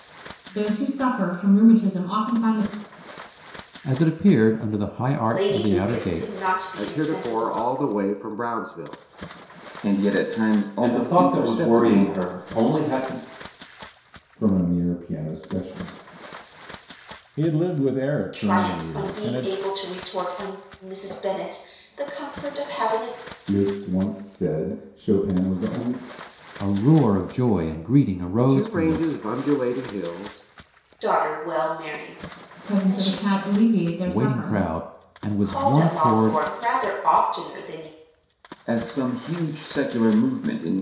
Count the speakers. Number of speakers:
8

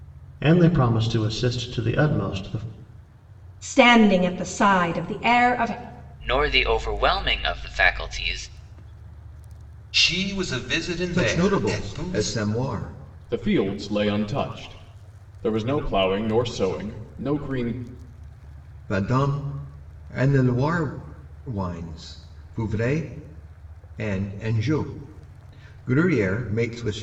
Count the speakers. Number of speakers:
6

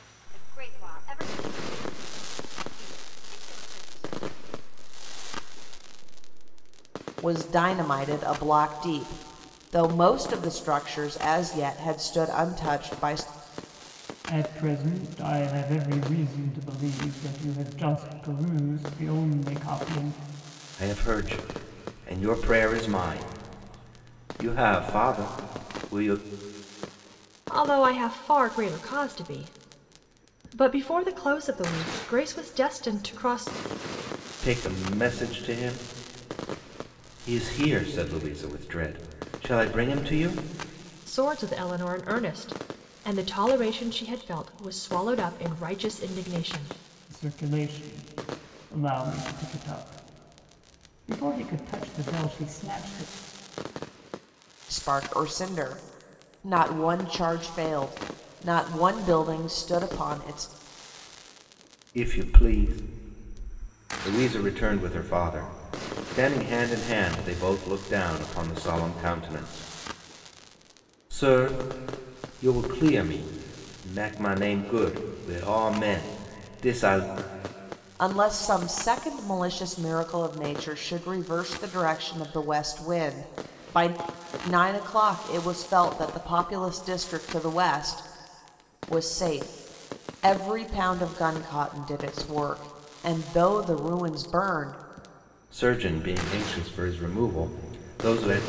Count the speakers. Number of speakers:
5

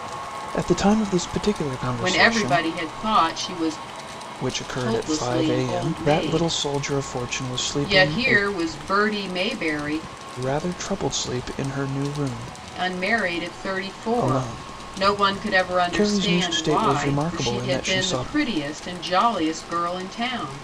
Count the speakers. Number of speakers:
2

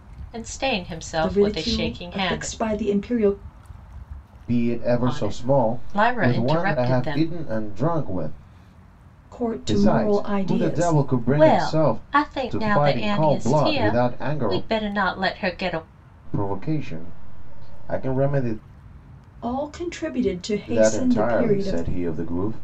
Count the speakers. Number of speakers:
3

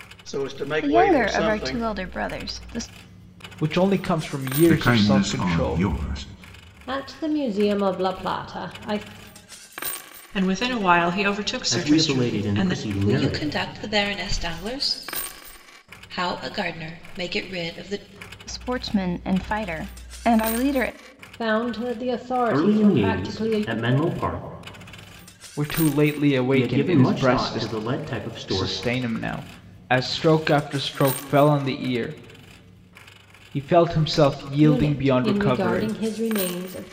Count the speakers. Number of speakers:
8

